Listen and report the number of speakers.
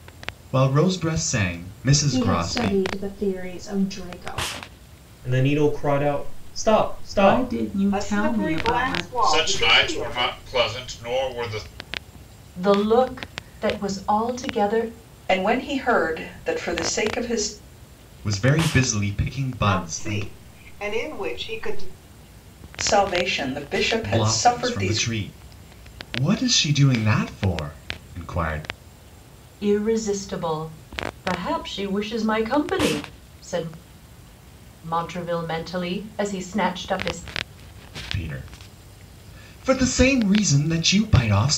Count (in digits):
8